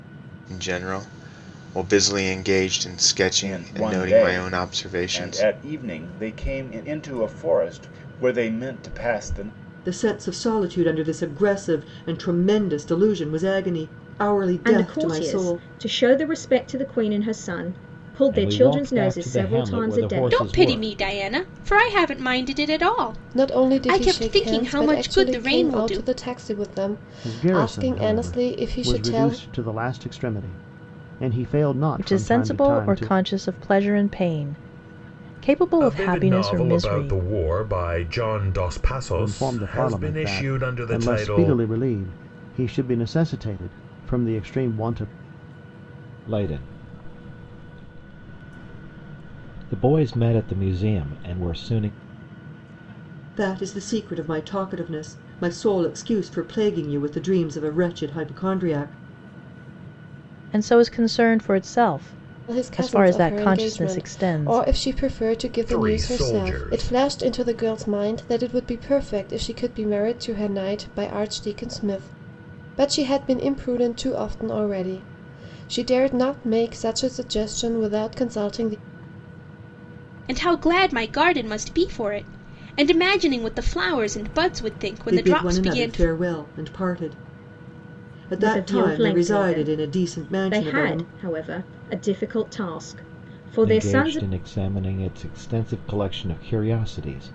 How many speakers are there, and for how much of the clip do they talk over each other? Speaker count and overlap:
ten, about 24%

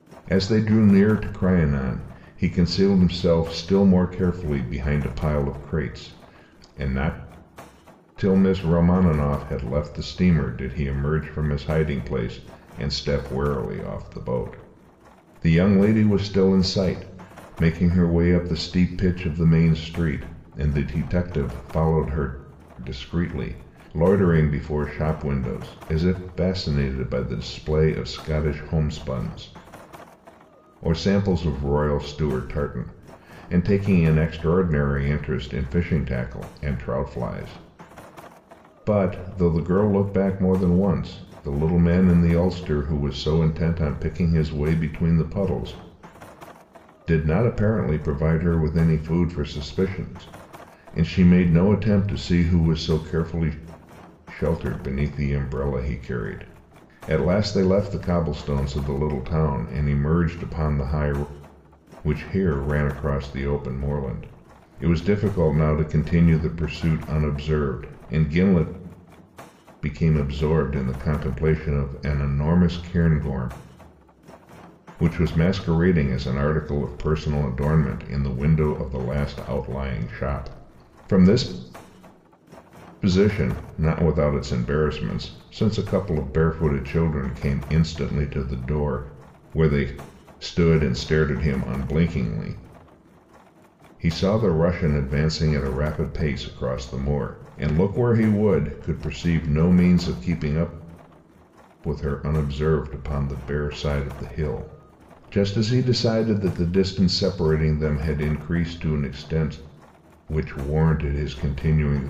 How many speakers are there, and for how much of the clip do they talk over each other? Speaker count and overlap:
one, no overlap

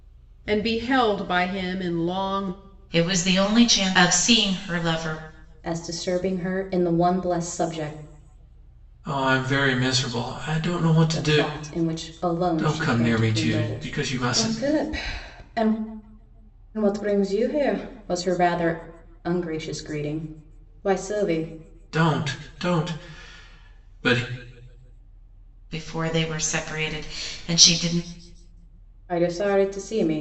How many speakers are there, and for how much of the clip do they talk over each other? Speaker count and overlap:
four, about 8%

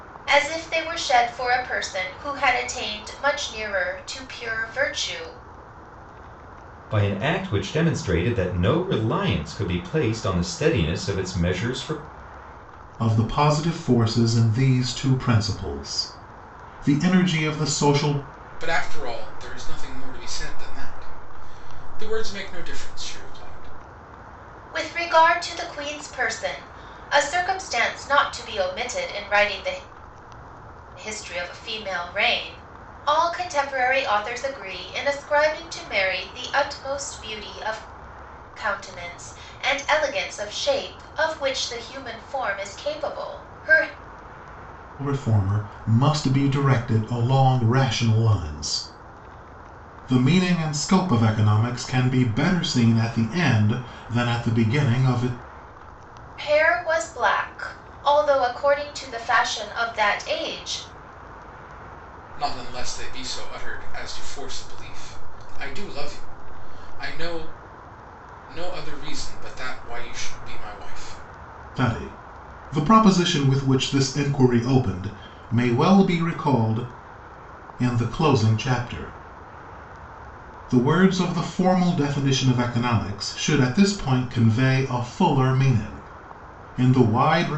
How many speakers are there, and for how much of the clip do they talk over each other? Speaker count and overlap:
four, no overlap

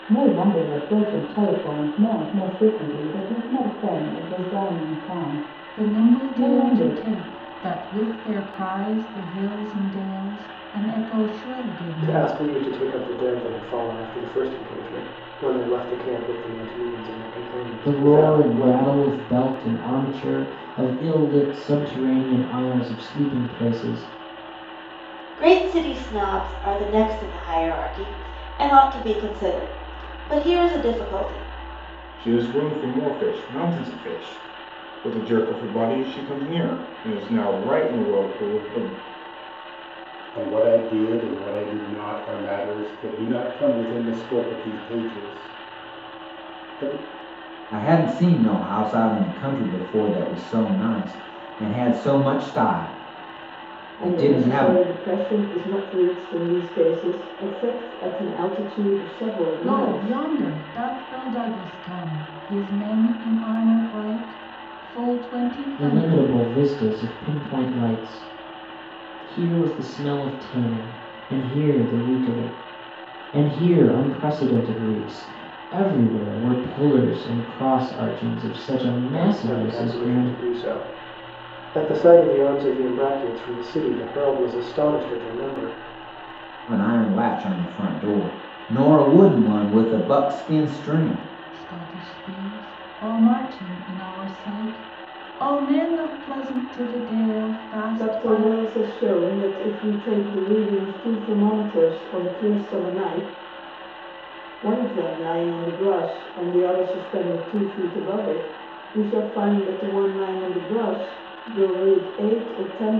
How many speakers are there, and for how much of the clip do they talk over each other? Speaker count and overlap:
nine, about 6%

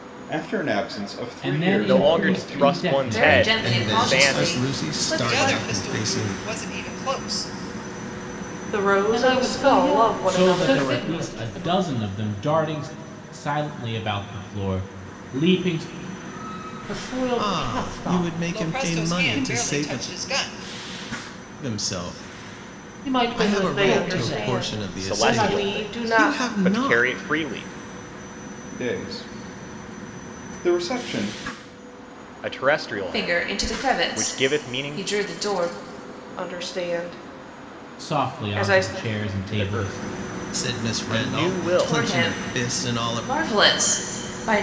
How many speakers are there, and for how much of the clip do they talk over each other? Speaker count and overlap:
eight, about 46%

